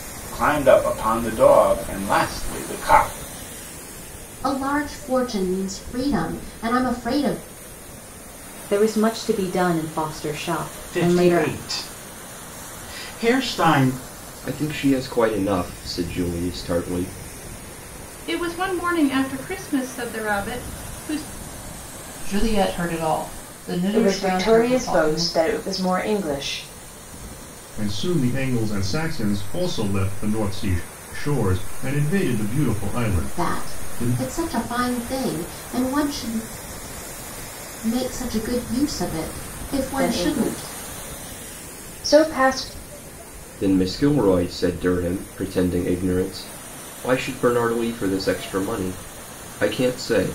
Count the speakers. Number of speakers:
9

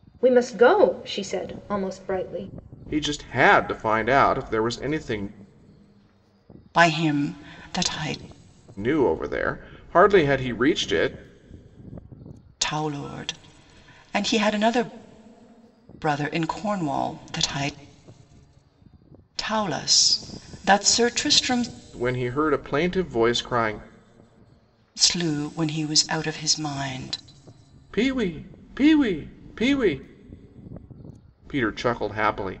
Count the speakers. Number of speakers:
3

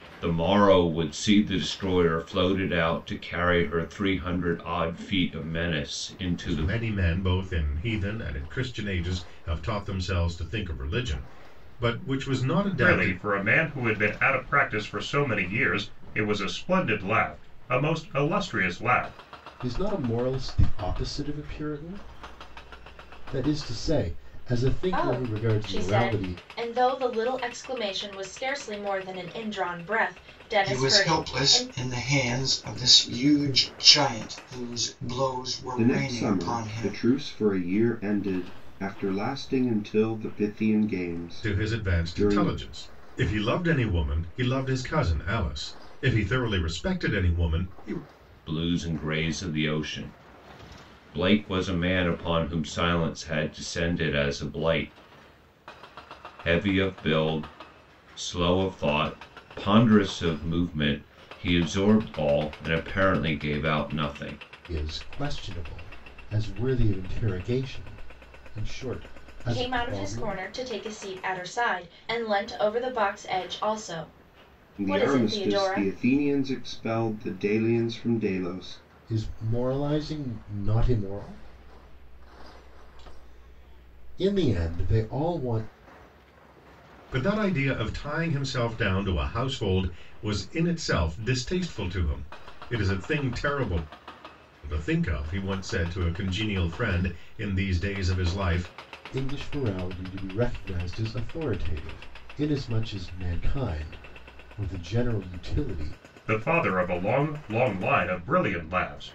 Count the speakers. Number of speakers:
7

